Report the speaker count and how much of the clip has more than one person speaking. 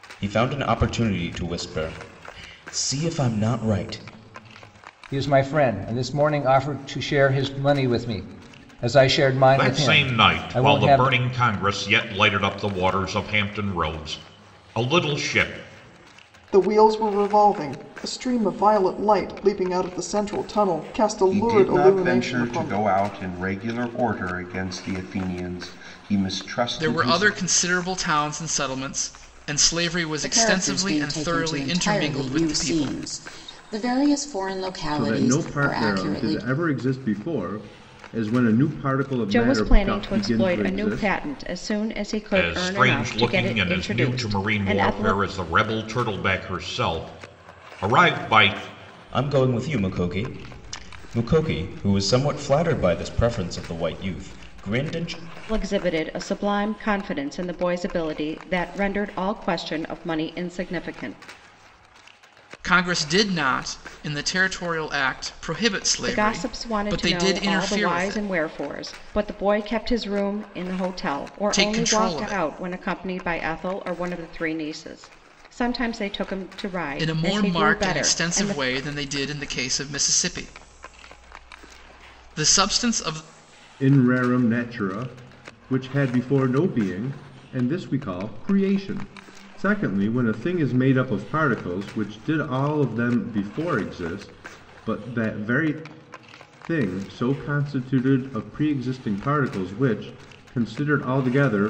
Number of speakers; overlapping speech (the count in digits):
9, about 18%